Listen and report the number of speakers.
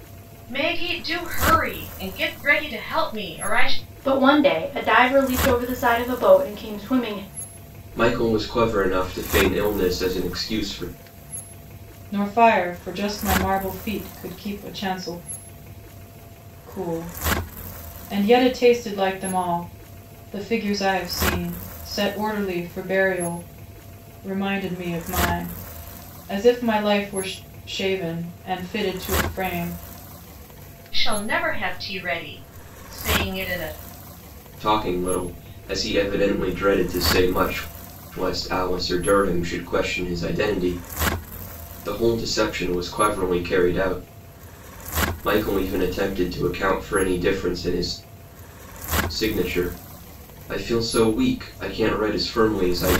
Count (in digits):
4